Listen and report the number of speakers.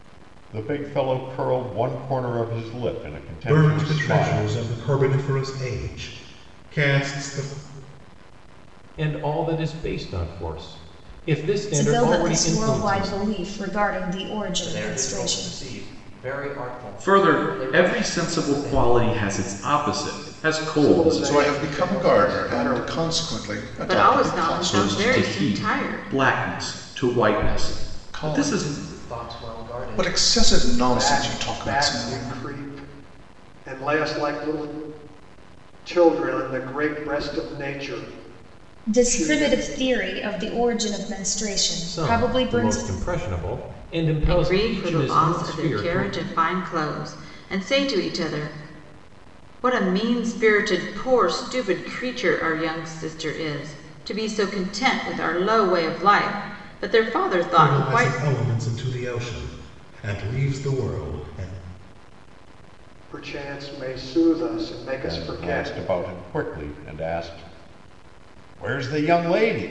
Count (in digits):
9